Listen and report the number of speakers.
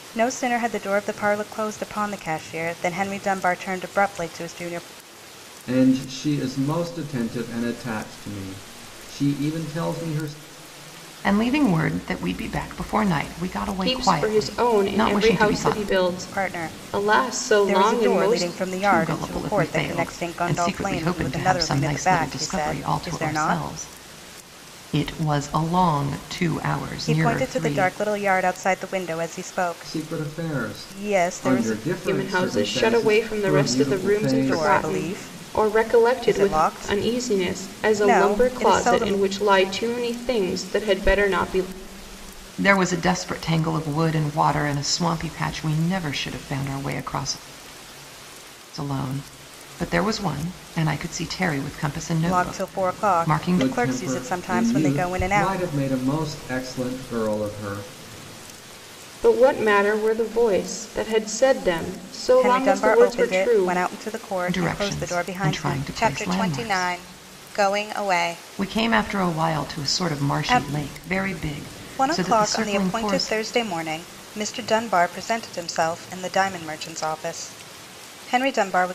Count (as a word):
four